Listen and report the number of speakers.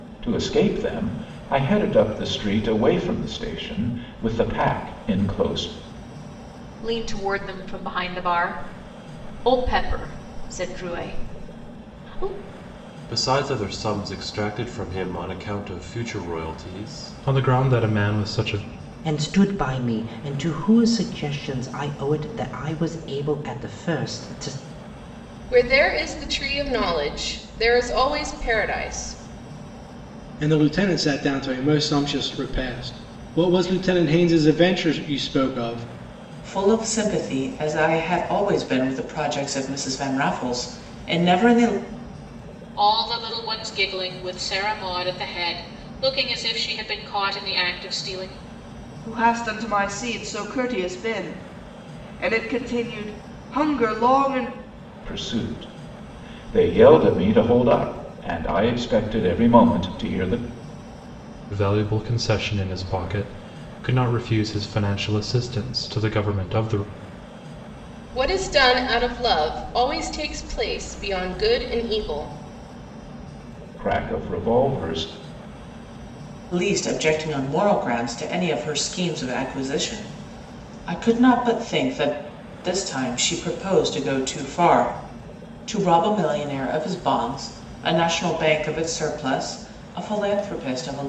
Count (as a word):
nine